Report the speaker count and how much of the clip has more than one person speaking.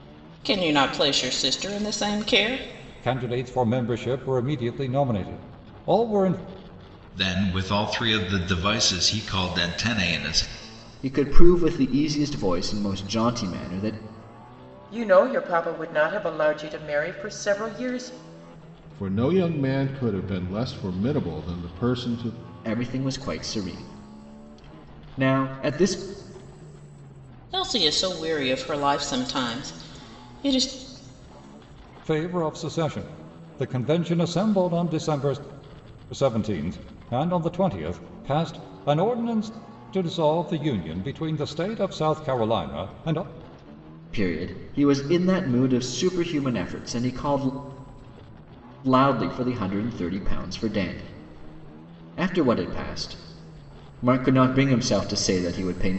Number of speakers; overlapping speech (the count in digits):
6, no overlap